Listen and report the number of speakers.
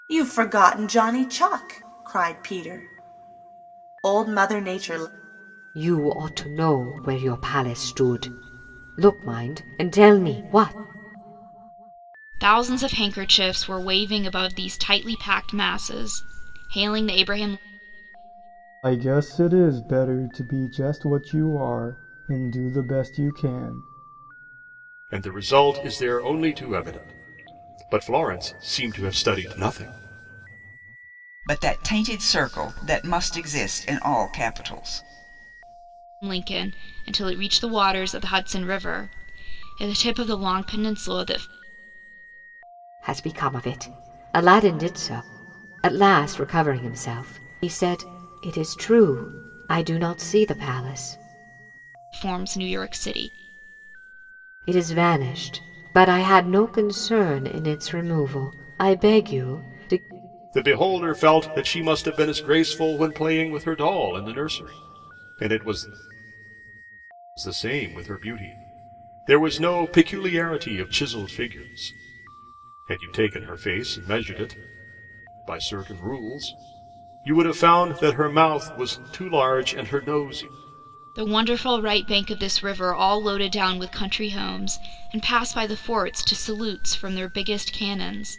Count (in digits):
6